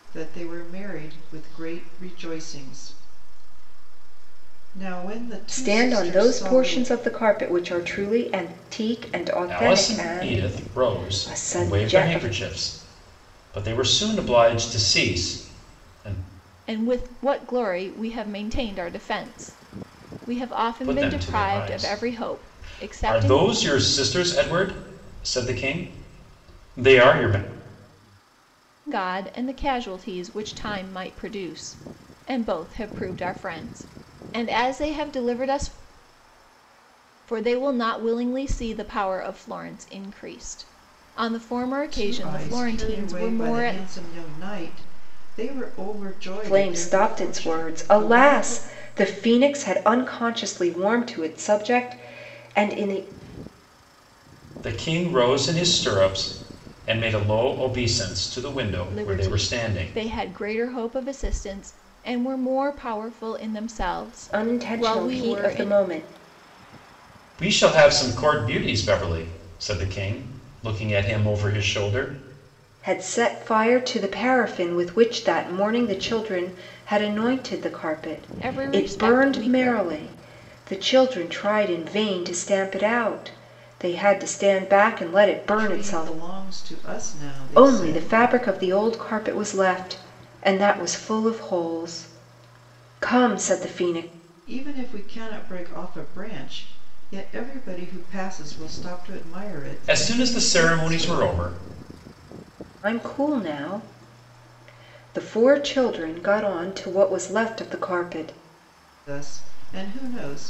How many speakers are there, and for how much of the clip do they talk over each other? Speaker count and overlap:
4, about 16%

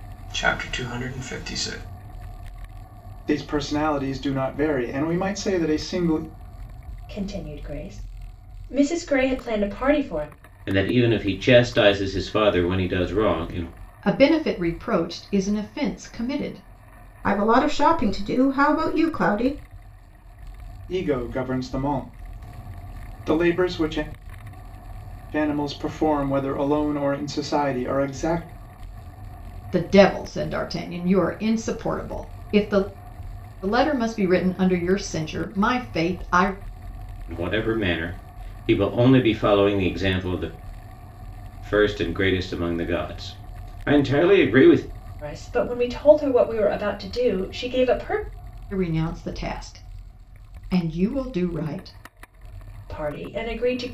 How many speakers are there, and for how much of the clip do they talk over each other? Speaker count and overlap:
6, no overlap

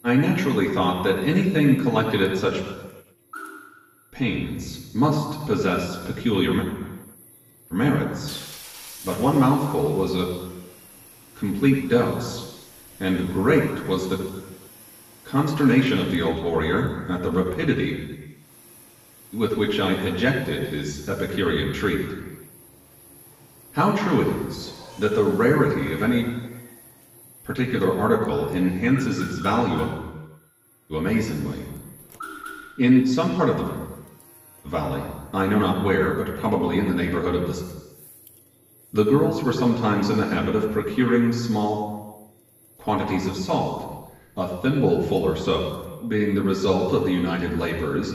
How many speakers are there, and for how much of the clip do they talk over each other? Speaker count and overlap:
1, no overlap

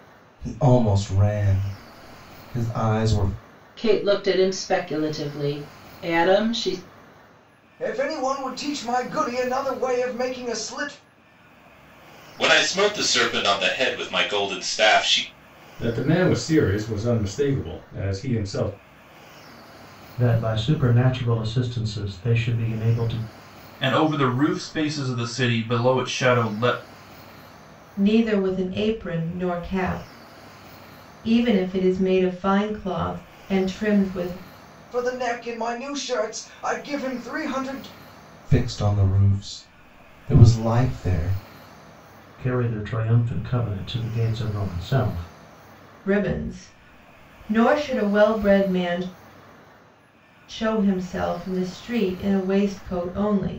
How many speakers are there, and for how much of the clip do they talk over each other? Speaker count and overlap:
8, no overlap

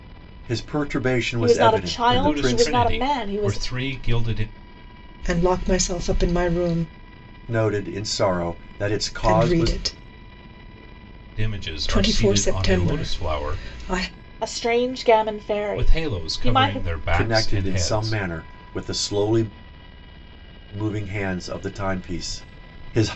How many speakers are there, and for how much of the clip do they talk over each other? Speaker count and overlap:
4, about 30%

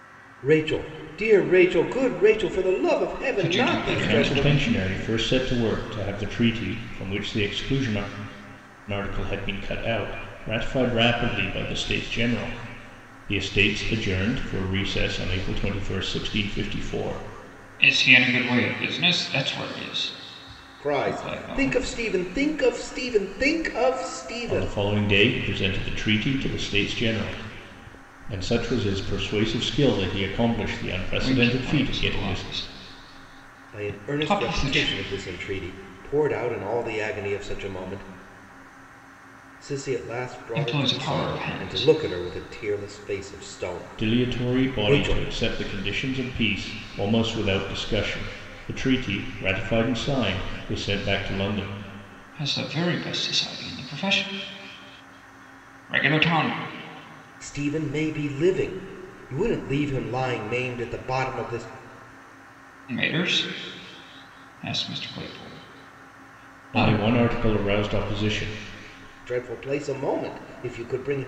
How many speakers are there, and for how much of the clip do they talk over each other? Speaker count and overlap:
3, about 12%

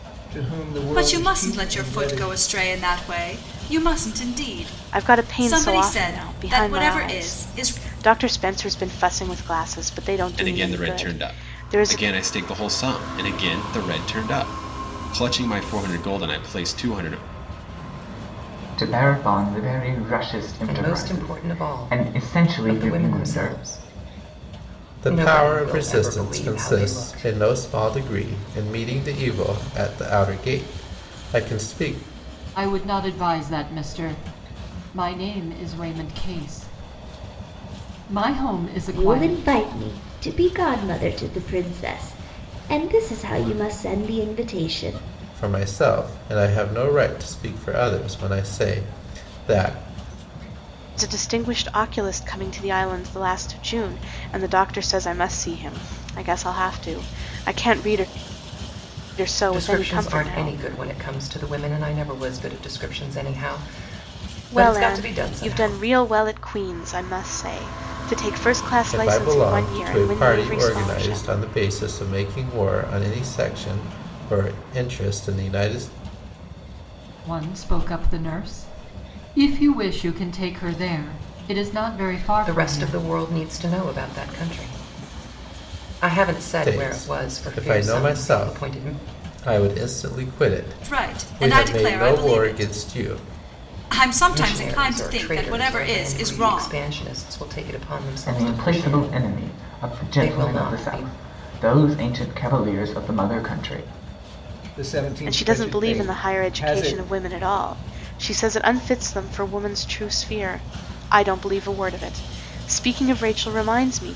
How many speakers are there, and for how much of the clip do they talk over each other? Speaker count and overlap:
9, about 26%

